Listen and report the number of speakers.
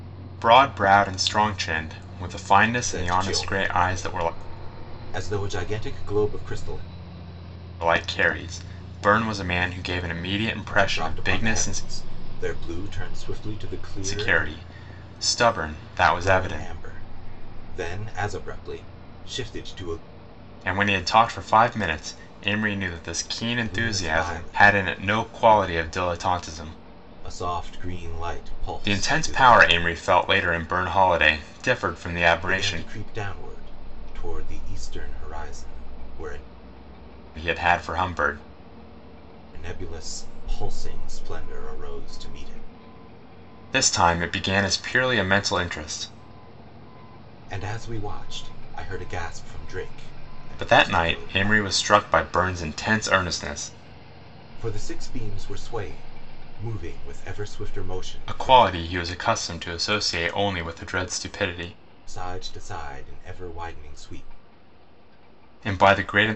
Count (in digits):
2